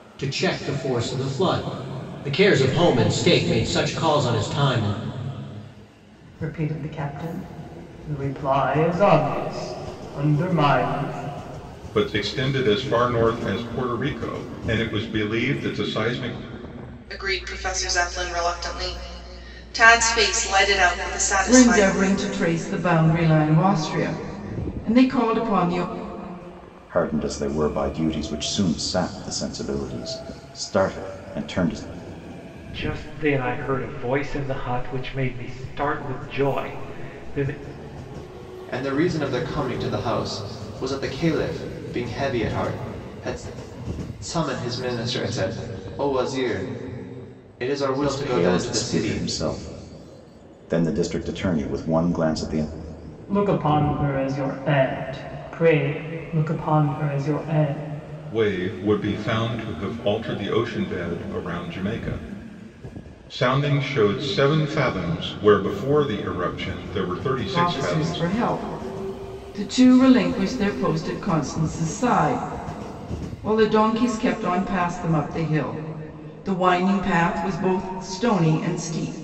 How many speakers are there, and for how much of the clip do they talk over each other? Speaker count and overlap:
8, about 3%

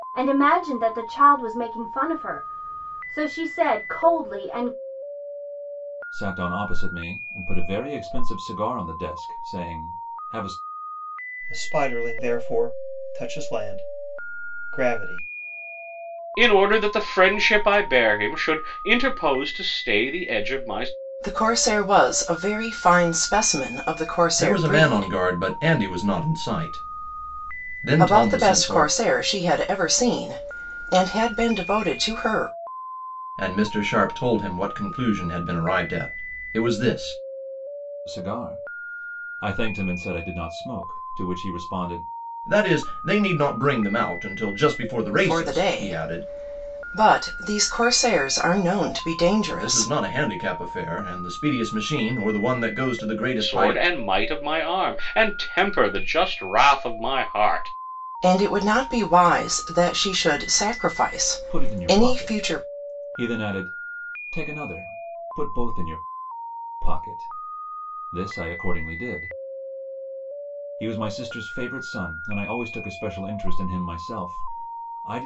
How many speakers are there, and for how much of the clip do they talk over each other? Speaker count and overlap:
6, about 7%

